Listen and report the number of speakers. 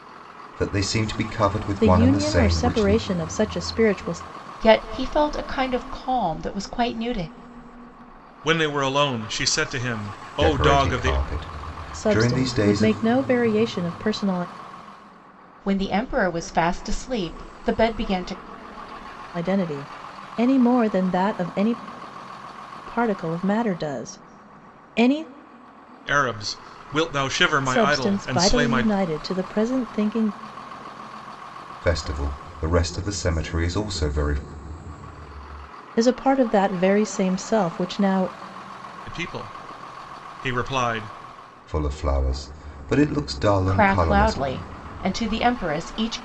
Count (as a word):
four